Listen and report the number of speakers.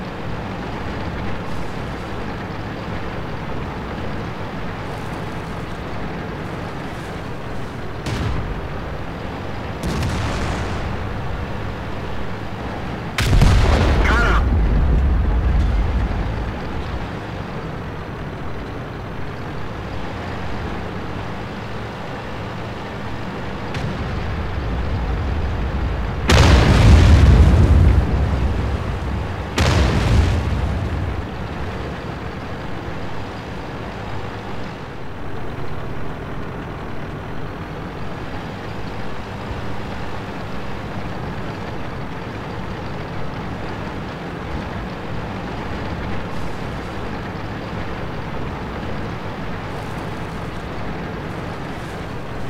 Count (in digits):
0